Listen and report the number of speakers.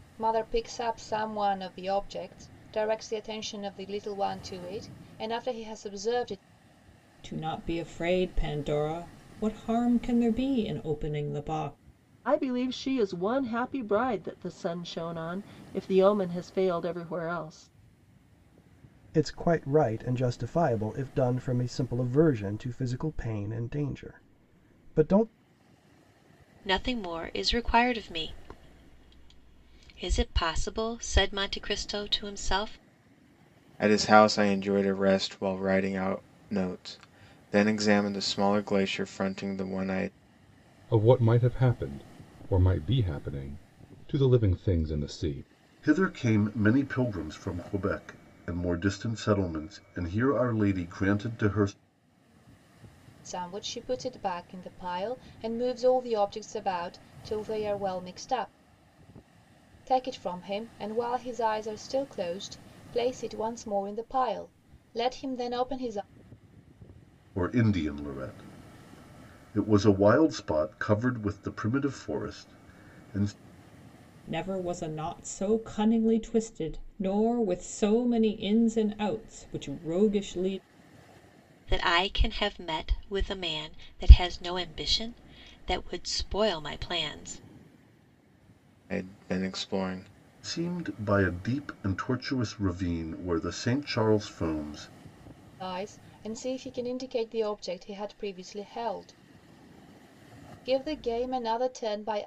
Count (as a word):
eight